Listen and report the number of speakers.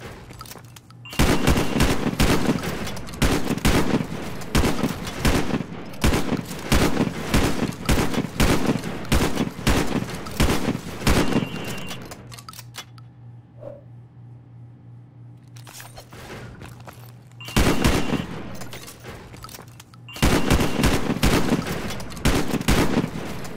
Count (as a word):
zero